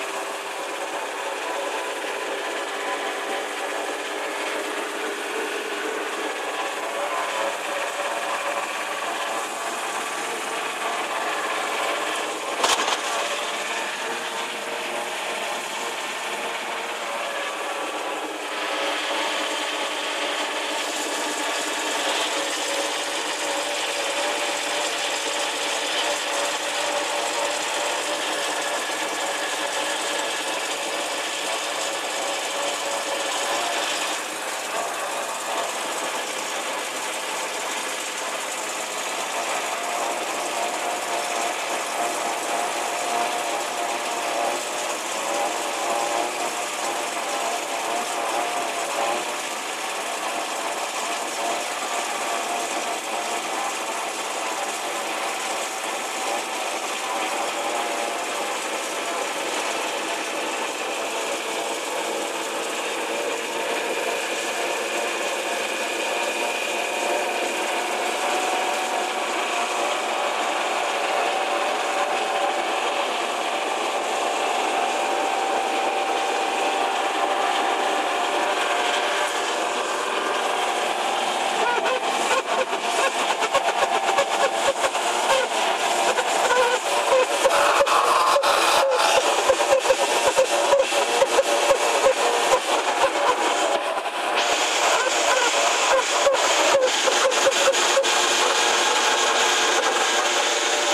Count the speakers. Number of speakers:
zero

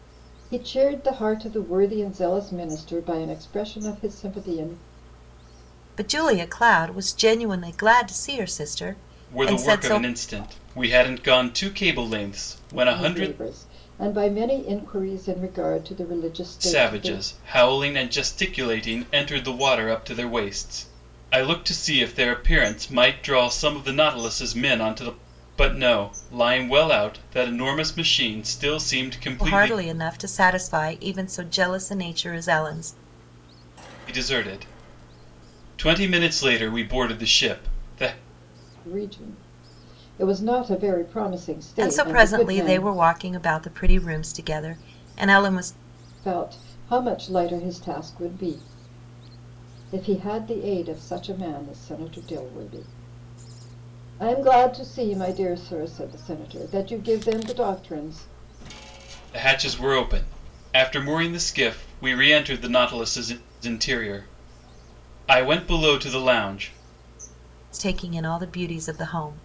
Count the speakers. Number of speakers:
three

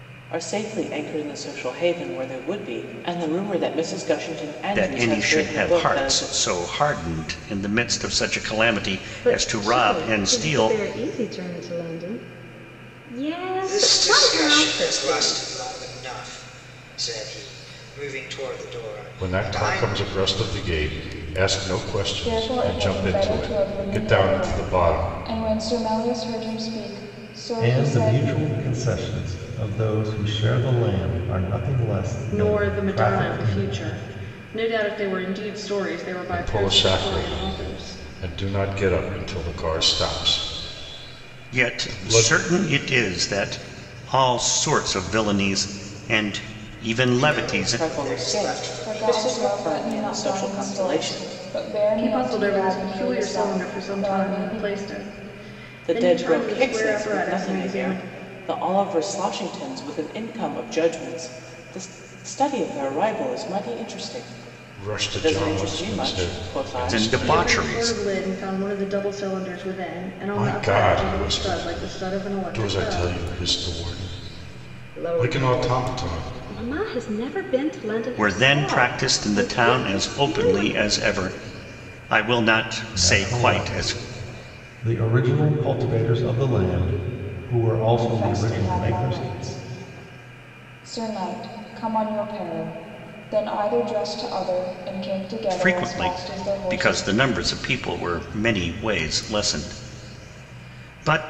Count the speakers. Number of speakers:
eight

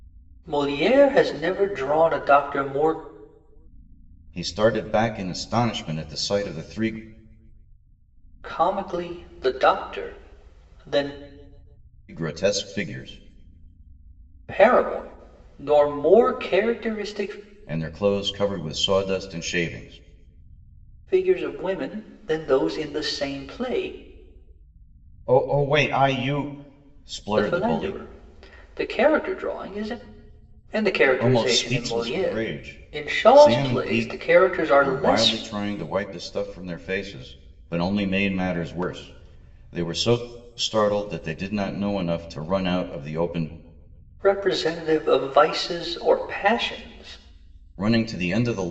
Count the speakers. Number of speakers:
two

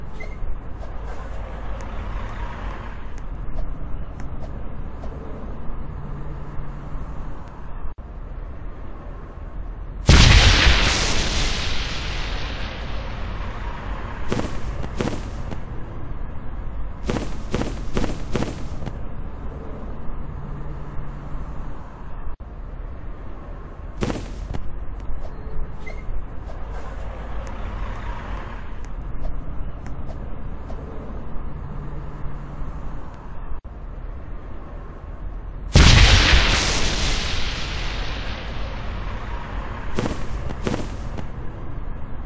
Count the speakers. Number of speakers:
zero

